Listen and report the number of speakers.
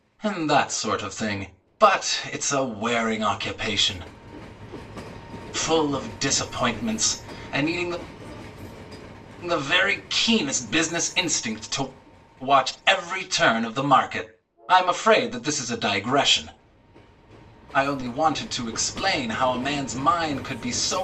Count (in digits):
1